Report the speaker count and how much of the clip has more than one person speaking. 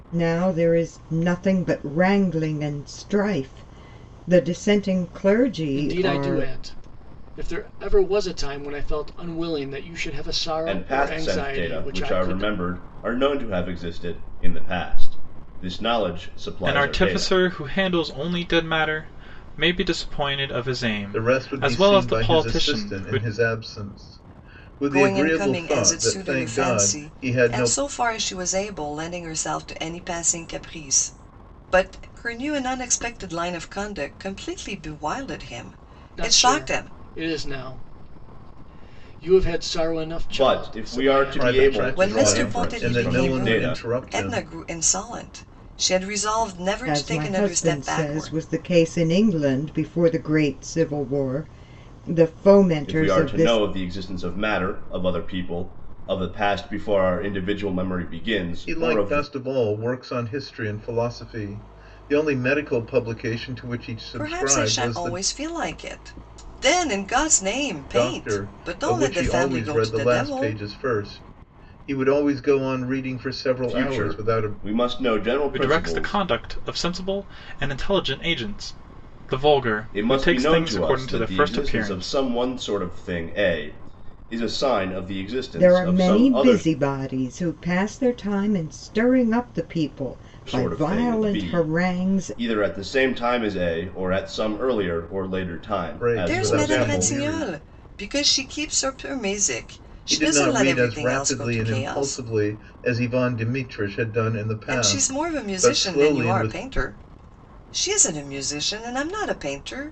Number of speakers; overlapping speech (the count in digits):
6, about 30%